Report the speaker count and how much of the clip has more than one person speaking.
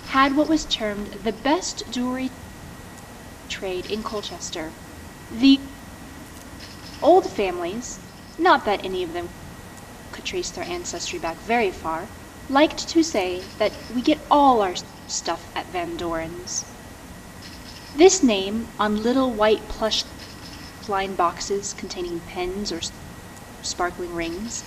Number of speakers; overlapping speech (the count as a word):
one, no overlap